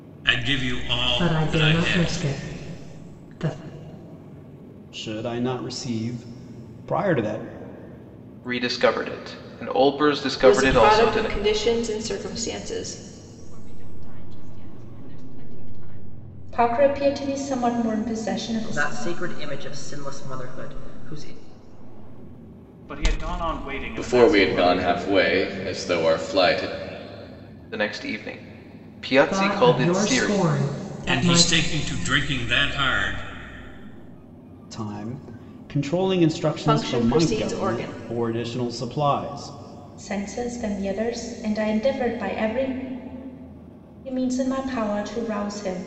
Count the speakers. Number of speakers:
10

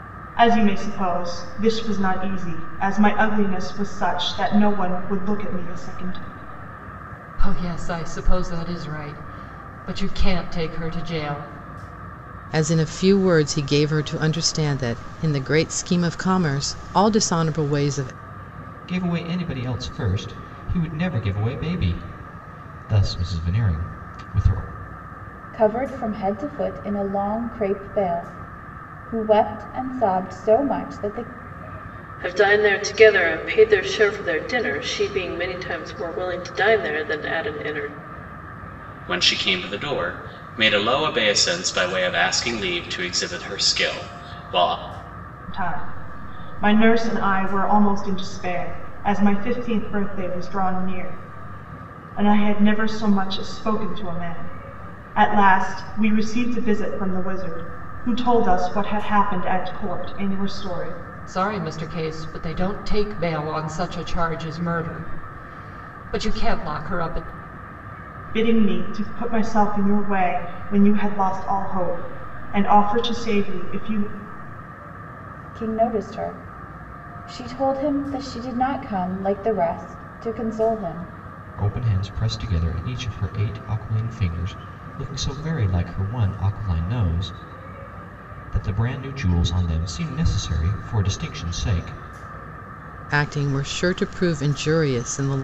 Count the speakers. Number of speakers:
7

